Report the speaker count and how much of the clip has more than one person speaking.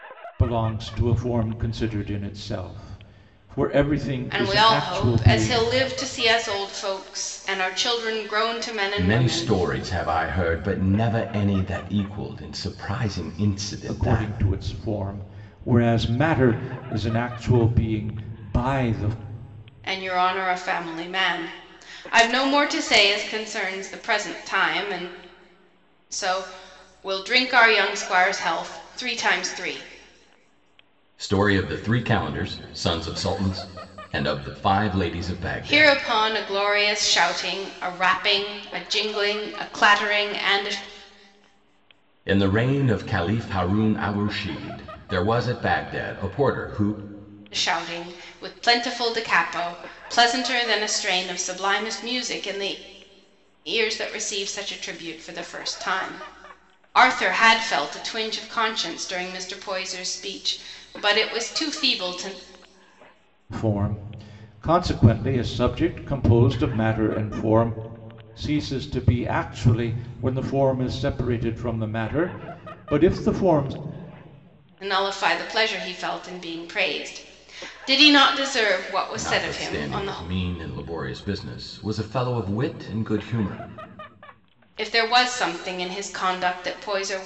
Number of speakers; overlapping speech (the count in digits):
3, about 5%